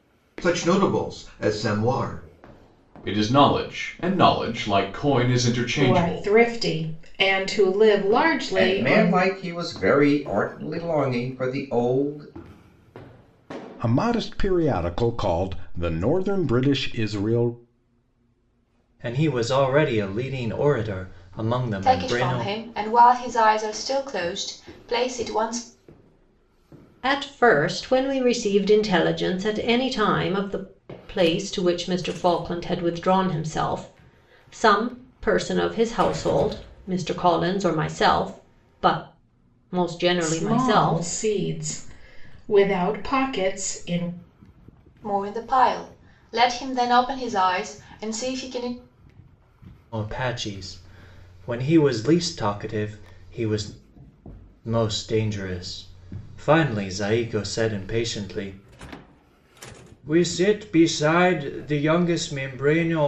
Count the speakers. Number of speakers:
8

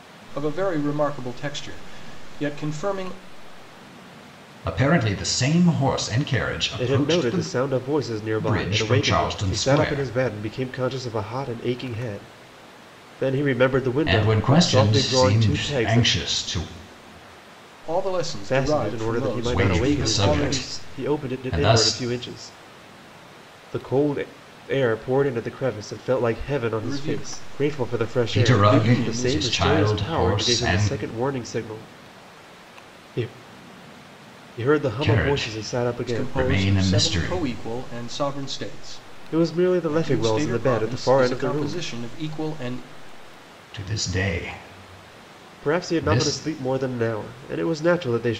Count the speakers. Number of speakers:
3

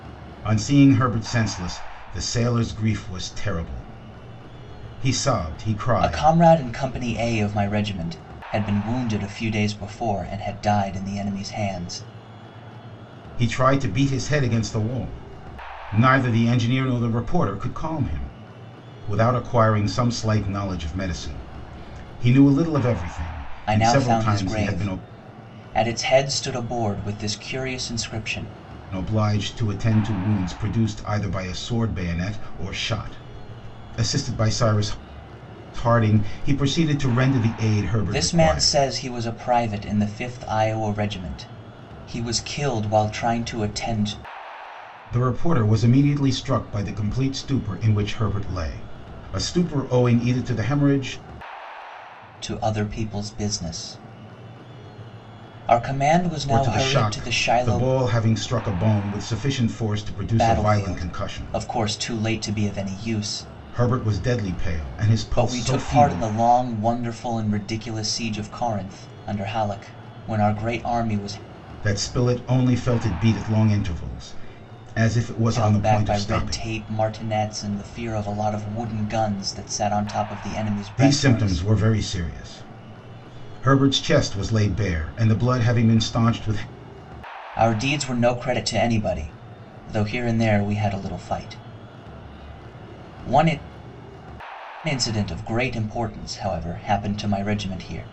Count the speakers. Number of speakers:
2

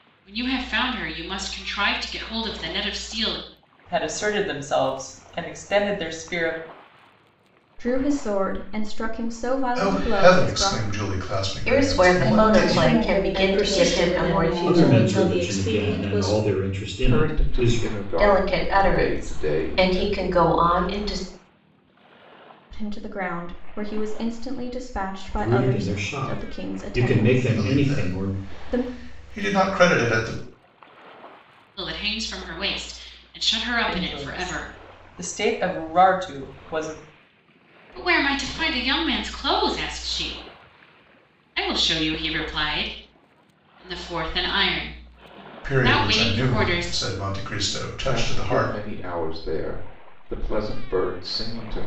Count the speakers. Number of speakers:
9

